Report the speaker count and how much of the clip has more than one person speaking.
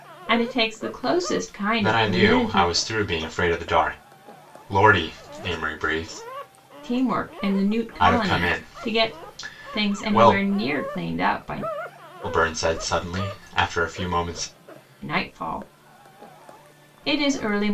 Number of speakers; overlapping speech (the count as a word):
two, about 16%